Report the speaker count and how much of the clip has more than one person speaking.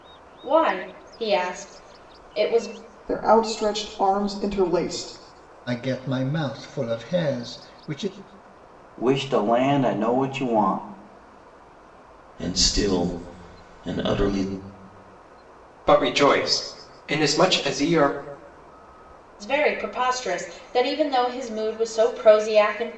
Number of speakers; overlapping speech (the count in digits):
6, no overlap